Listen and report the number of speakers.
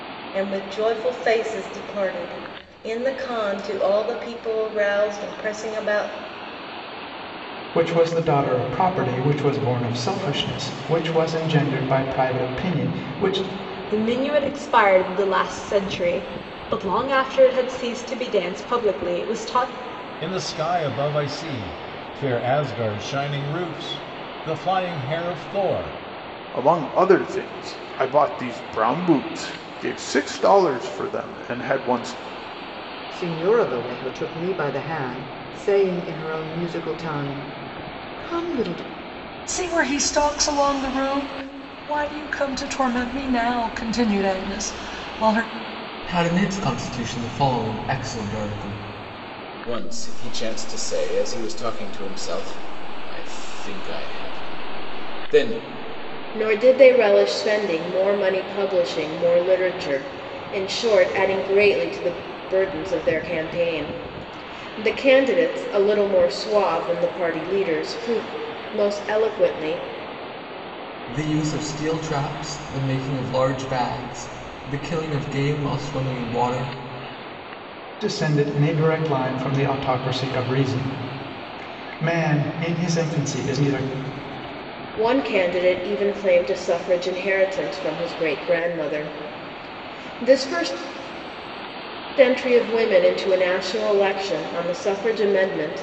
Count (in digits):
10